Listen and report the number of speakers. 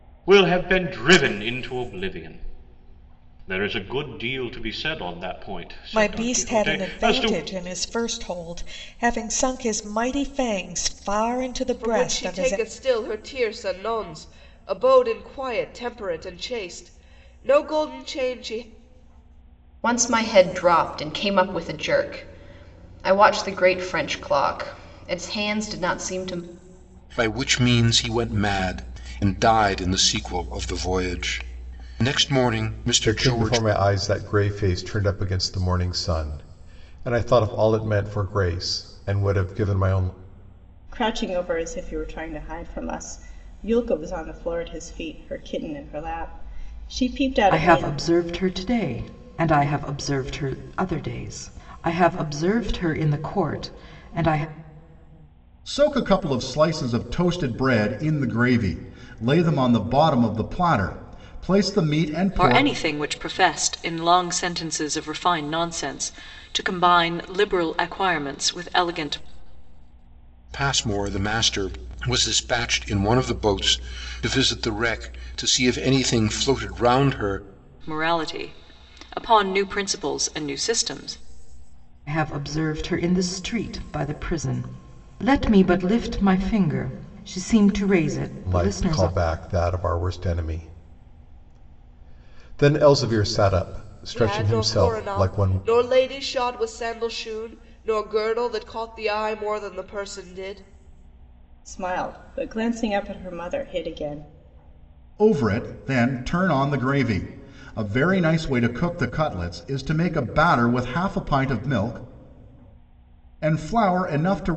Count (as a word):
ten